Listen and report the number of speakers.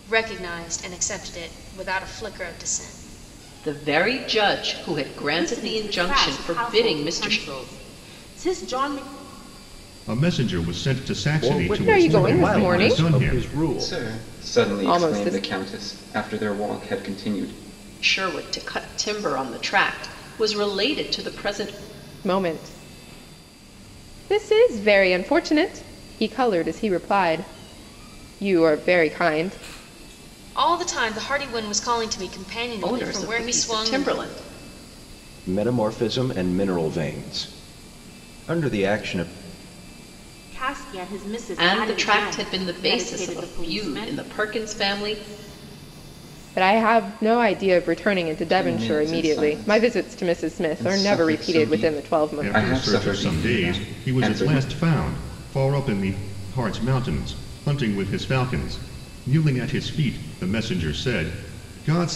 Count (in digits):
7